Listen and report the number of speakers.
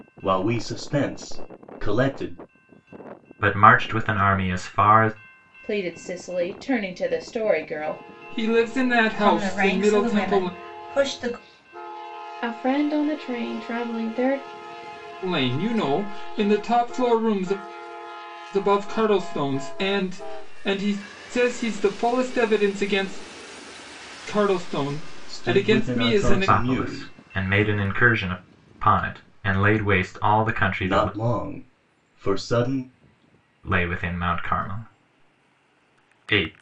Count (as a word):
six